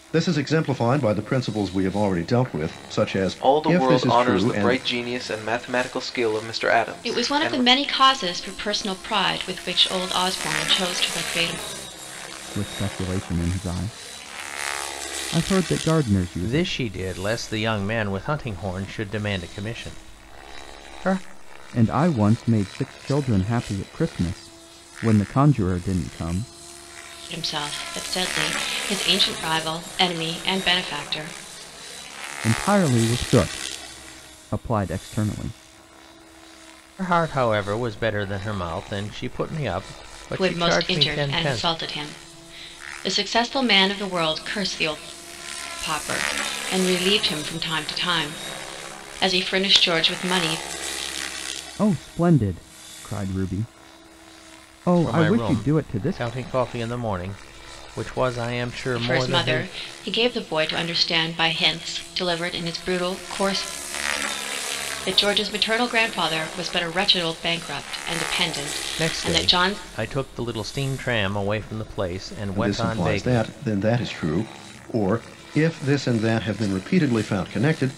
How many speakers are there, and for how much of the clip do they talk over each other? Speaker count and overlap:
5, about 10%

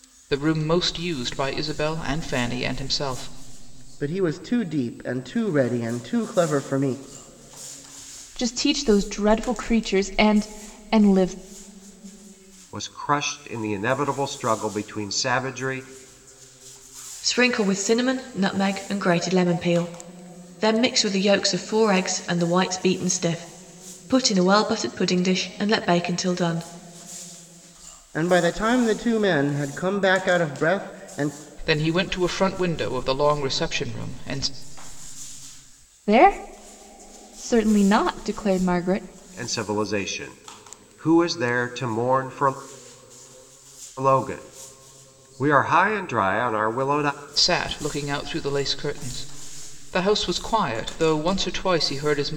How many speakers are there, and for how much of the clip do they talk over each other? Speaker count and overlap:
5, no overlap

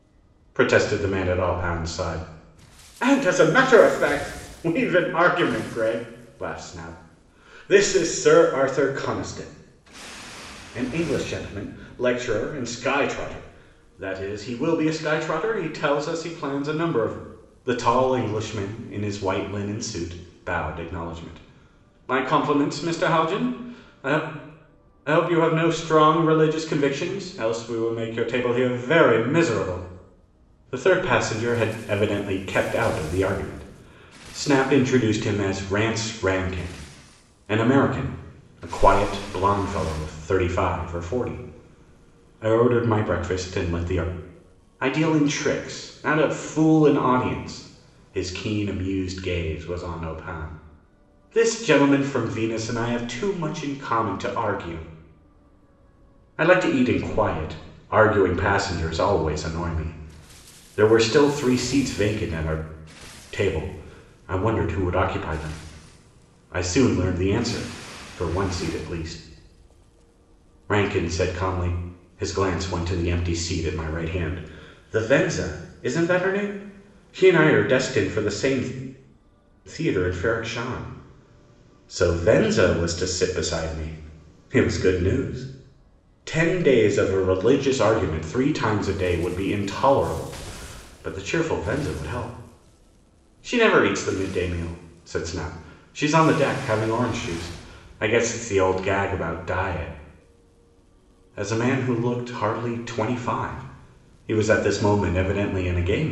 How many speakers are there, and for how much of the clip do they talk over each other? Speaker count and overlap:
1, no overlap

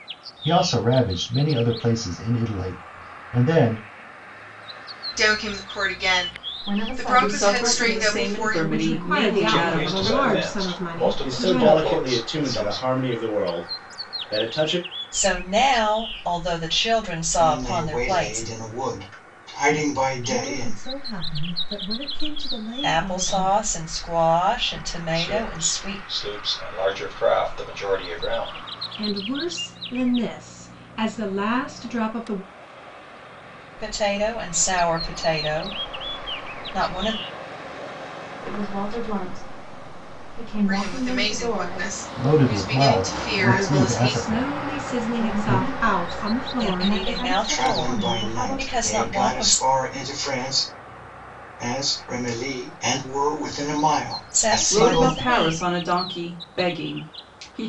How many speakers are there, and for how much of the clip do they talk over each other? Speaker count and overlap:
10, about 34%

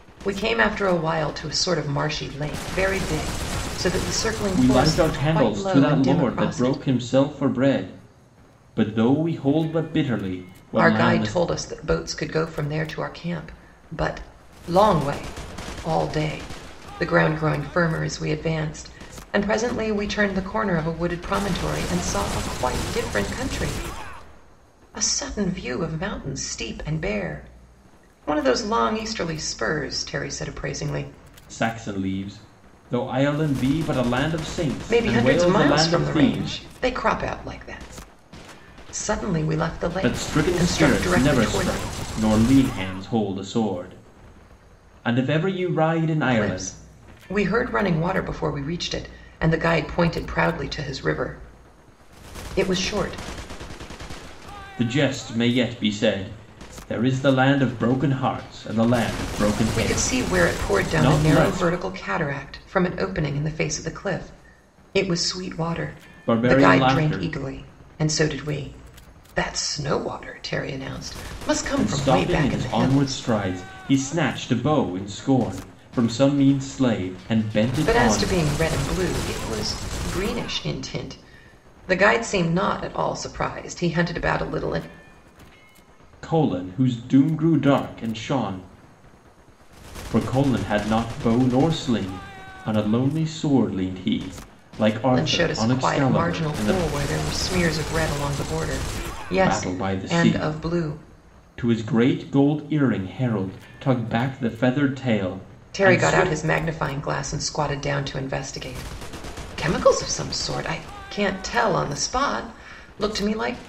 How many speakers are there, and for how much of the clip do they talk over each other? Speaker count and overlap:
2, about 14%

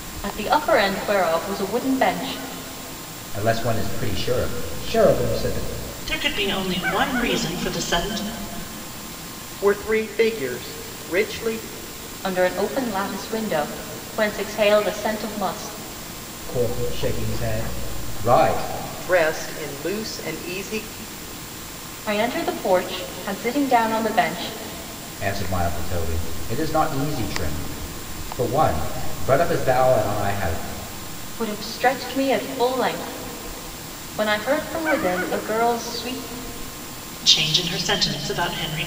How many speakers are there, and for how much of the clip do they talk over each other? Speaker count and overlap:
4, no overlap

